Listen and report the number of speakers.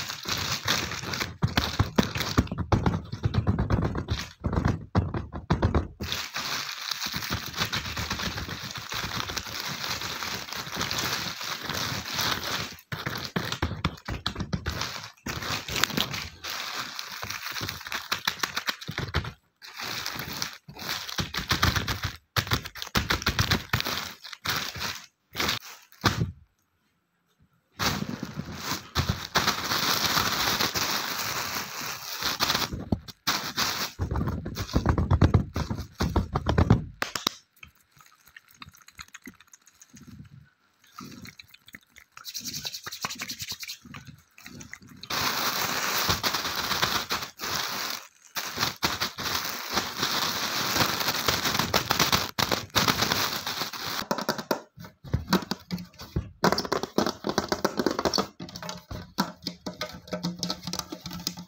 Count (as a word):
zero